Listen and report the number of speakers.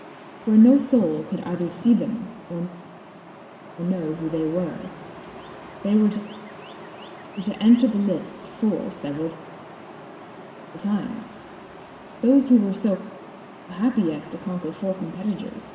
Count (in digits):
1